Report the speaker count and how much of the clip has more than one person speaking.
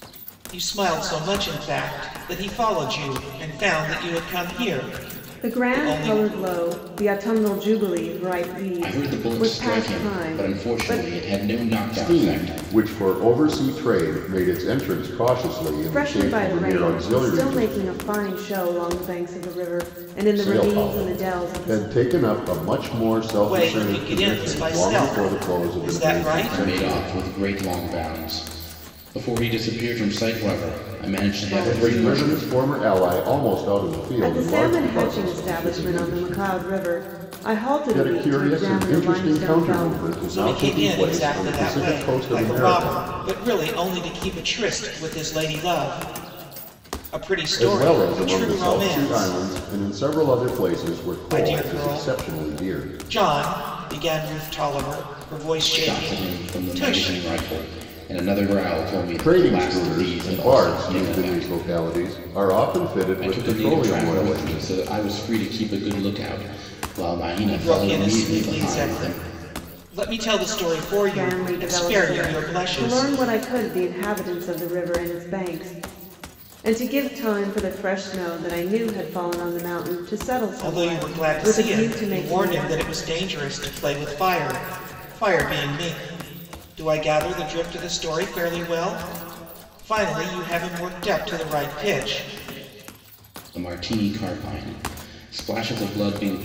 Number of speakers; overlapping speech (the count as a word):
four, about 35%